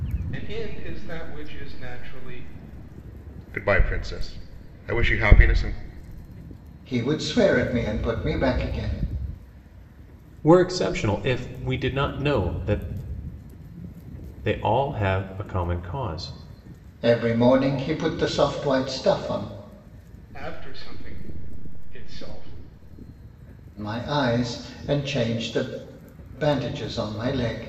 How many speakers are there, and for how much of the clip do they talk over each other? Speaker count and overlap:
4, no overlap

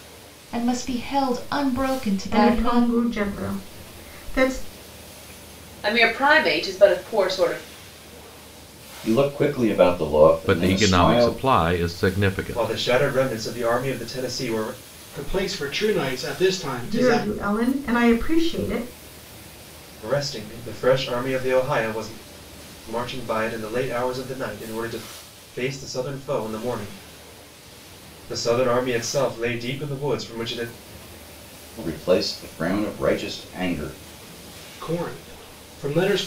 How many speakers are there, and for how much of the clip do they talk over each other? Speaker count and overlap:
7, about 7%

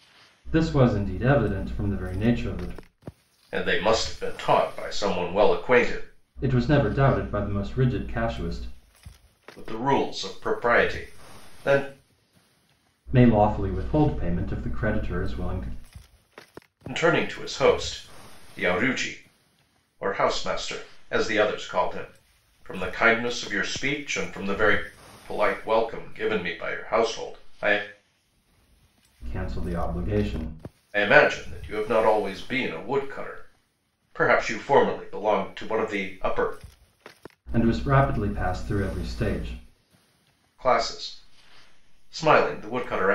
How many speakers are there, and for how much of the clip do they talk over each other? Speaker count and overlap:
2, no overlap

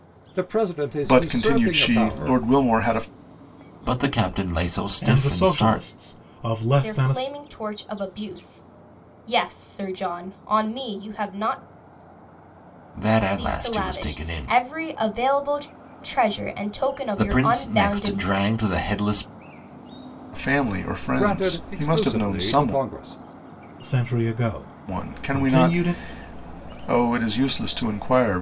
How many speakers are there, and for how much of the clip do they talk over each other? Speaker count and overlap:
5, about 28%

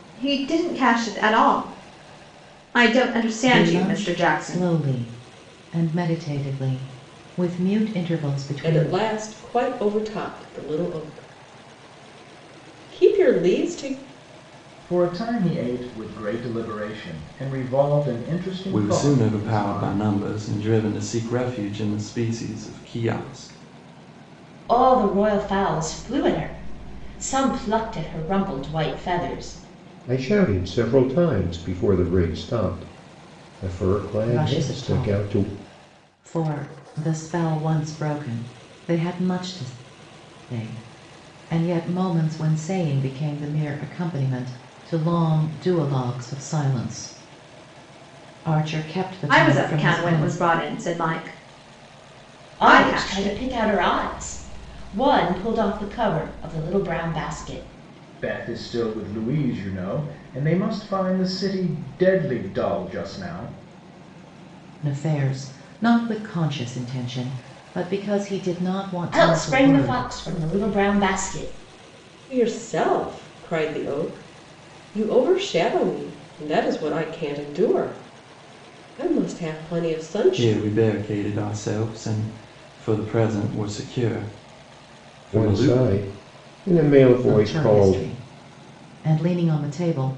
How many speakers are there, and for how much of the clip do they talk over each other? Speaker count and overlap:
7, about 10%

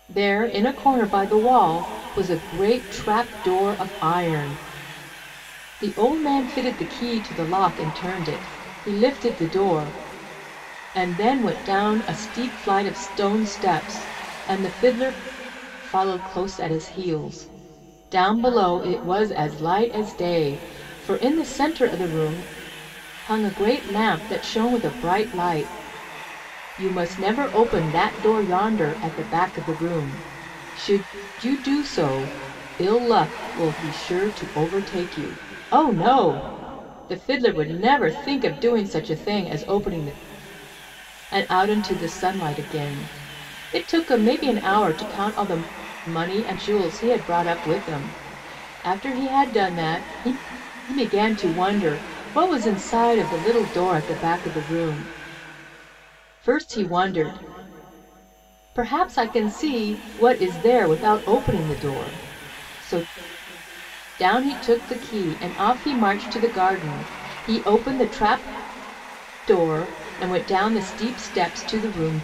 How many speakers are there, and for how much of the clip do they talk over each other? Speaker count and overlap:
1, no overlap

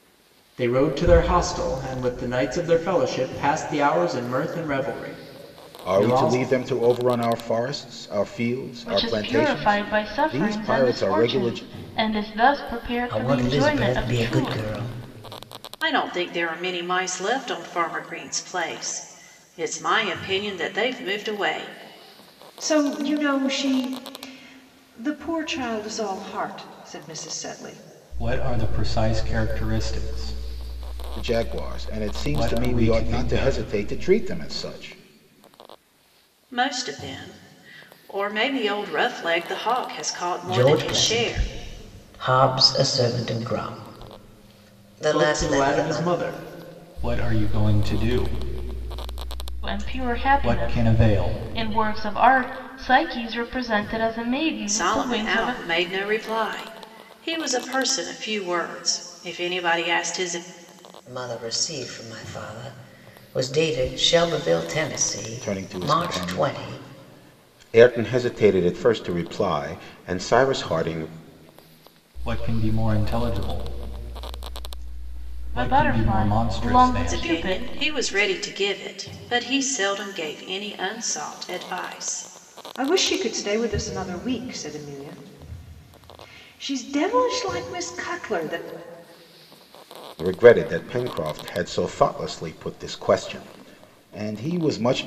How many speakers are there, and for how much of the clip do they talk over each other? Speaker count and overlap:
7, about 17%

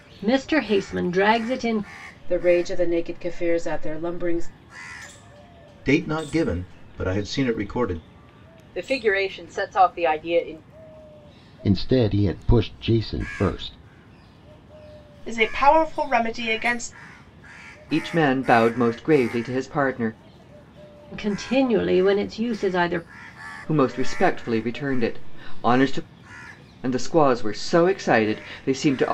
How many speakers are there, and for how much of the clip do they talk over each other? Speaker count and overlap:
7, no overlap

